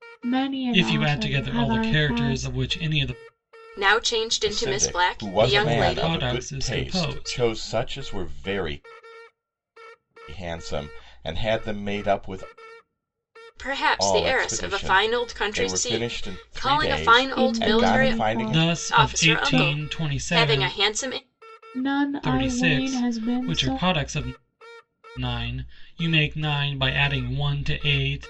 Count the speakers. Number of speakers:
4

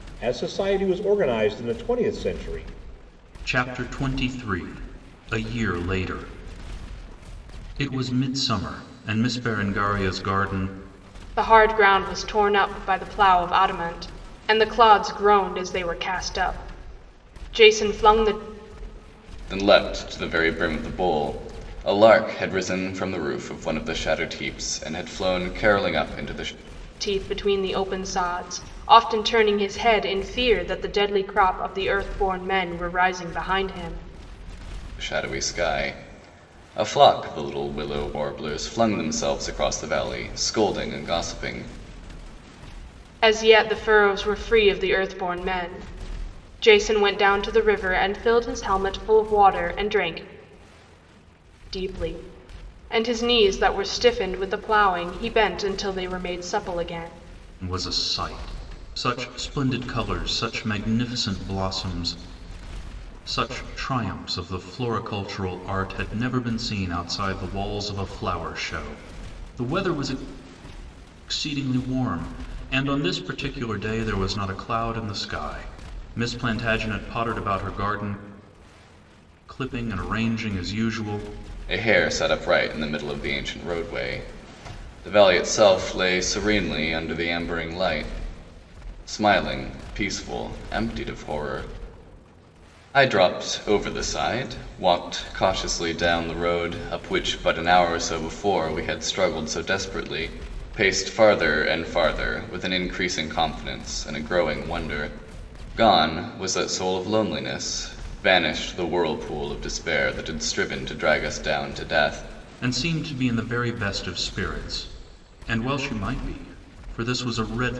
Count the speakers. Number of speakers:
4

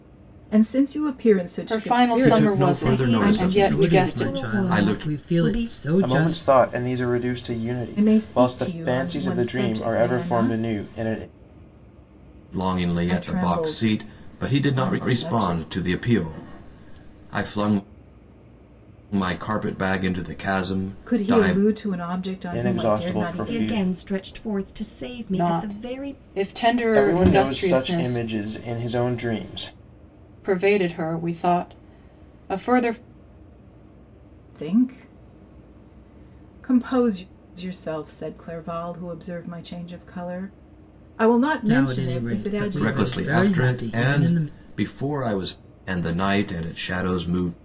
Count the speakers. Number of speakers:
6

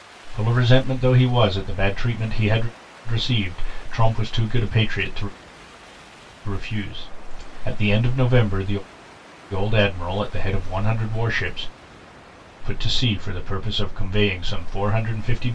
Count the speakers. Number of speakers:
1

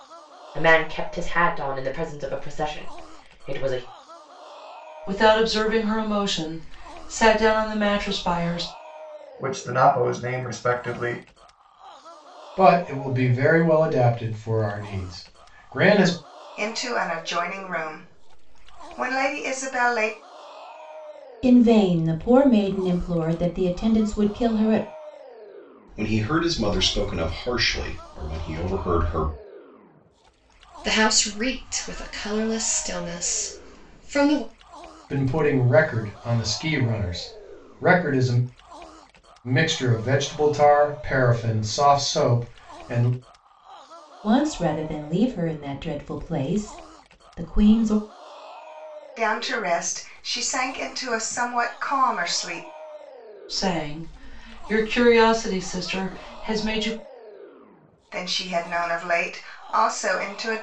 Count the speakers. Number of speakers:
8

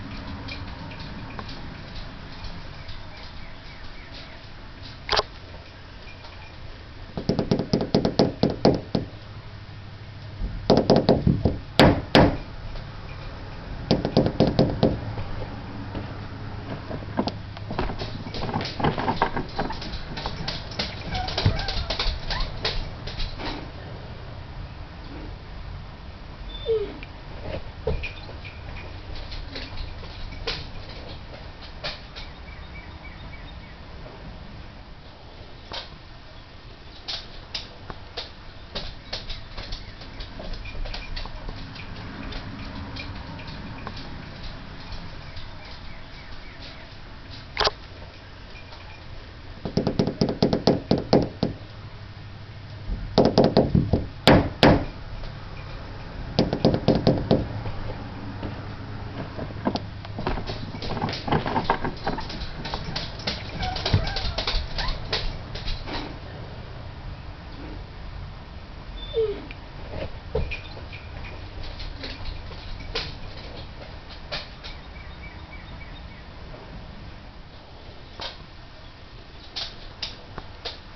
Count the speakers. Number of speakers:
0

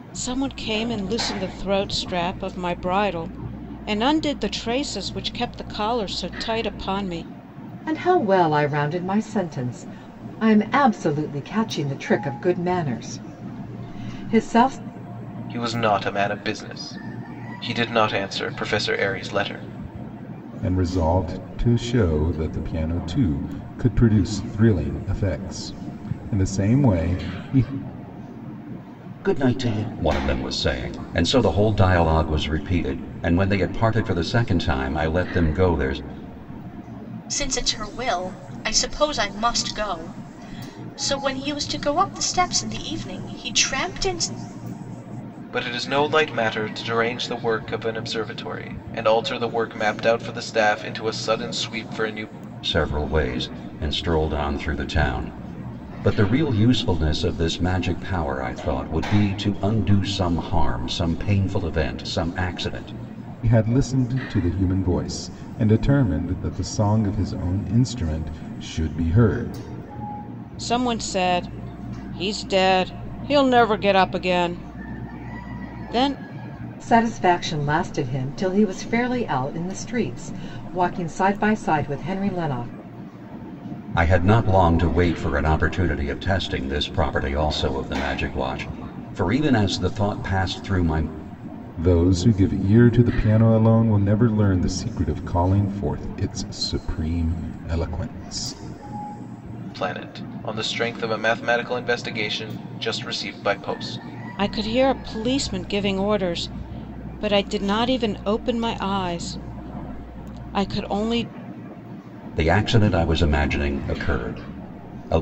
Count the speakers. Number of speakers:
6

